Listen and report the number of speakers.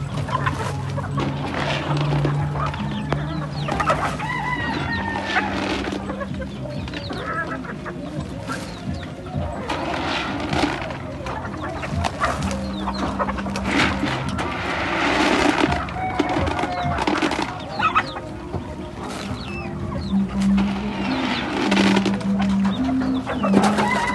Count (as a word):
zero